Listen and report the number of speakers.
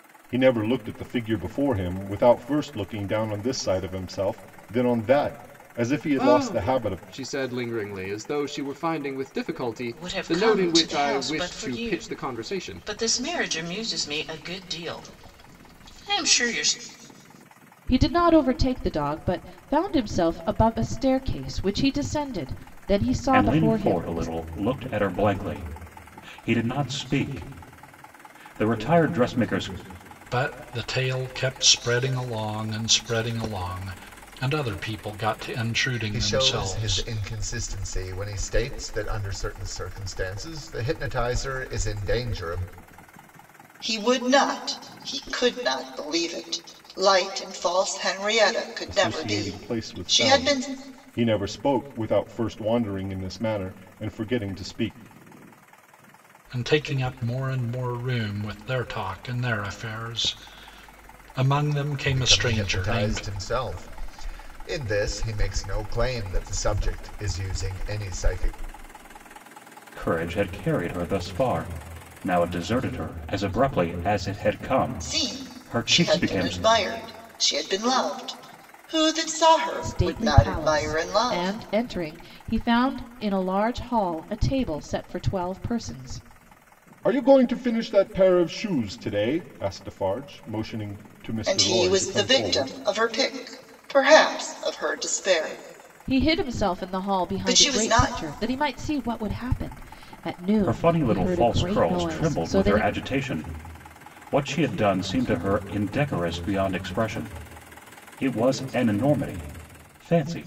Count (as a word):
eight